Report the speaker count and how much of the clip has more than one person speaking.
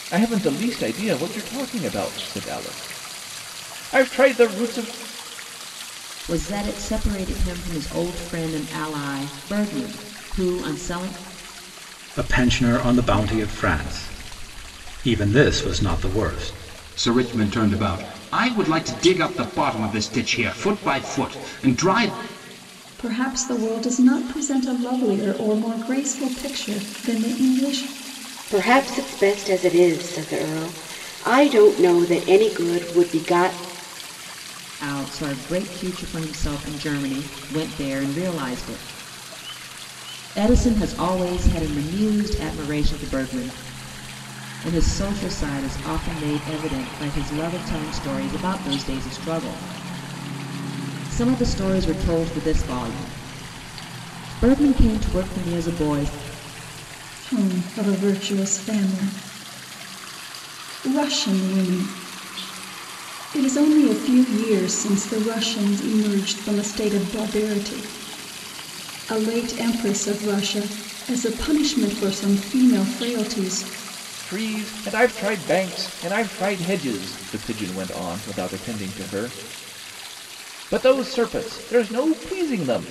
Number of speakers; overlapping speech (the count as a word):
six, no overlap